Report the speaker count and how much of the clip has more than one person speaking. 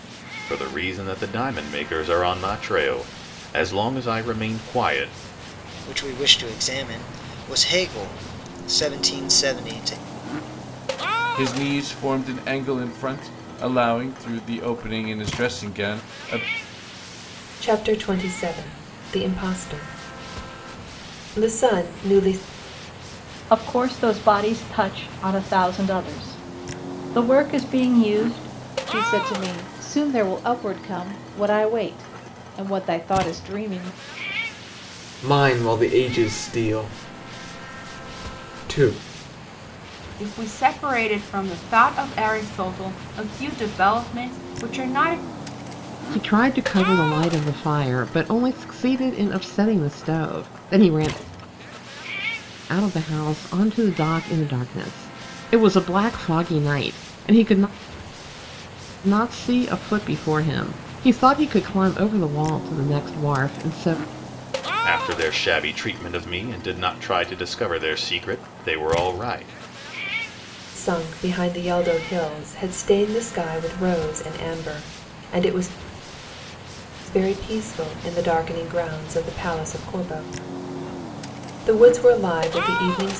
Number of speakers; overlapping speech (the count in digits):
9, no overlap